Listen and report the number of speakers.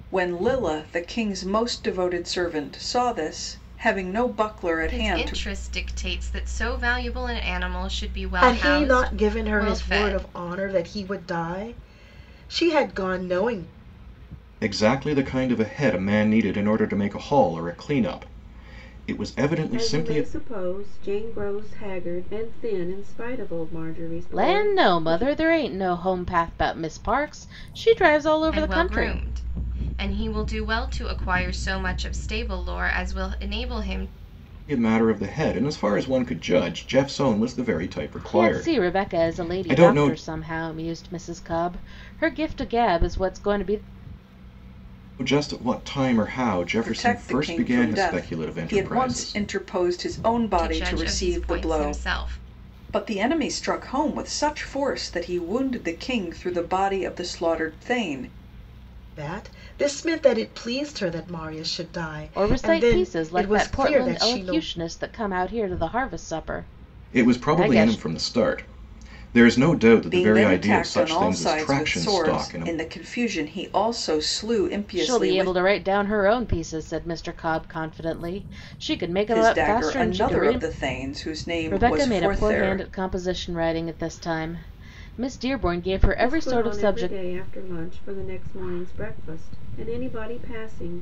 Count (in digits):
6